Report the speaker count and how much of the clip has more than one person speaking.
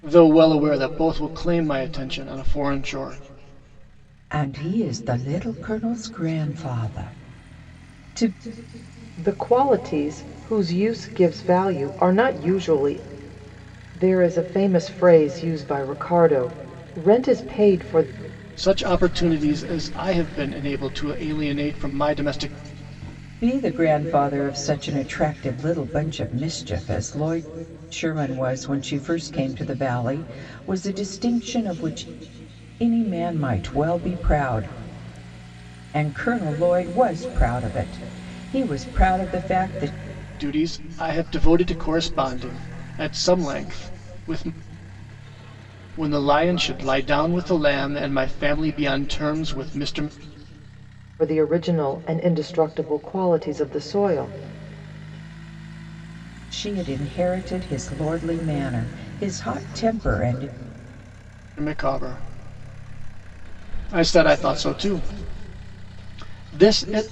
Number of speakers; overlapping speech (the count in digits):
3, no overlap